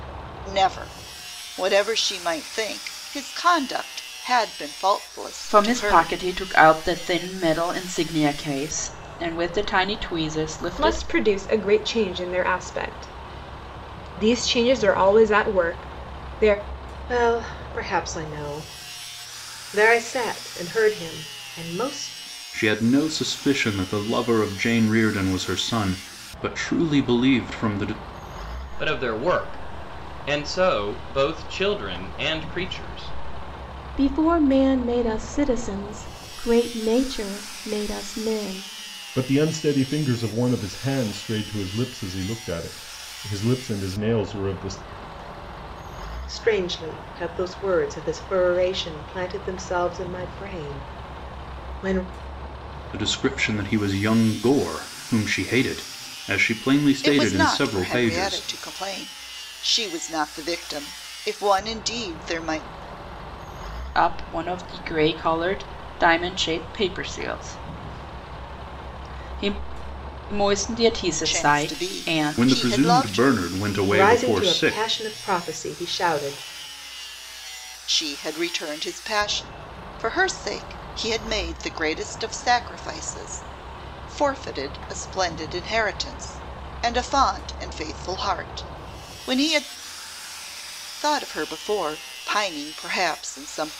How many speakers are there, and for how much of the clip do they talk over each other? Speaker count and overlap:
eight, about 6%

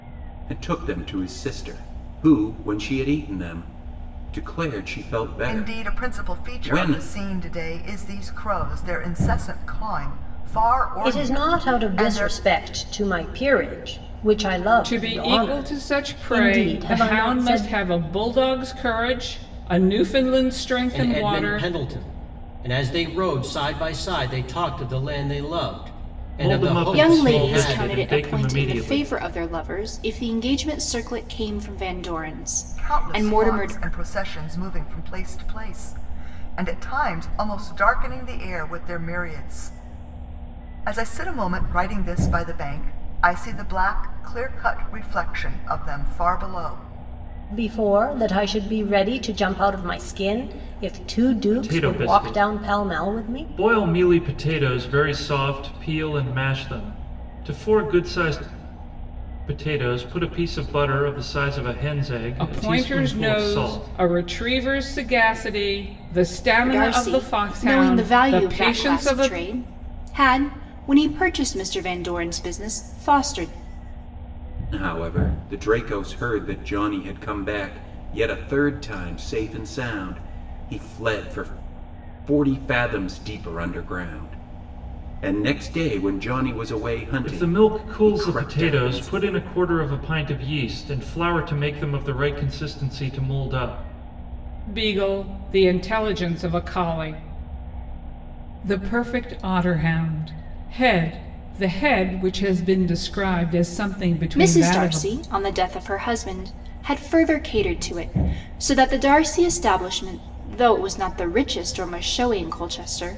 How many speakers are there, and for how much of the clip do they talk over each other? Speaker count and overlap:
seven, about 17%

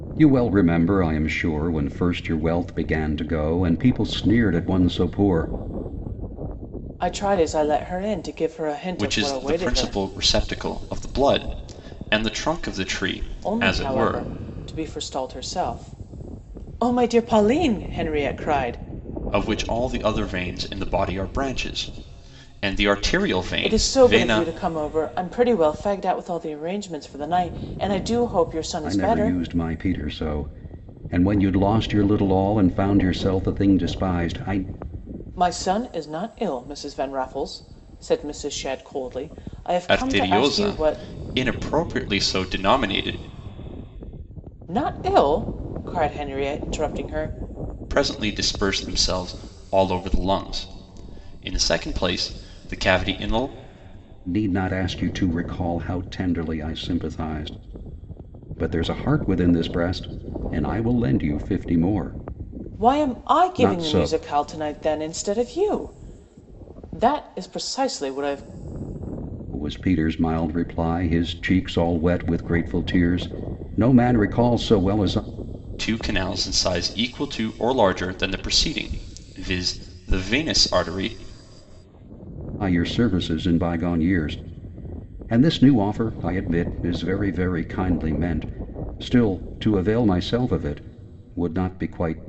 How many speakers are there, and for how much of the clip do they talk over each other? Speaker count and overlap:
three, about 6%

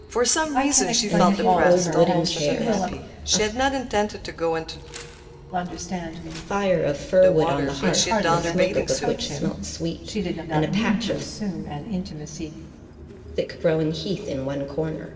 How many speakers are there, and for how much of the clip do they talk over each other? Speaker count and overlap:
three, about 51%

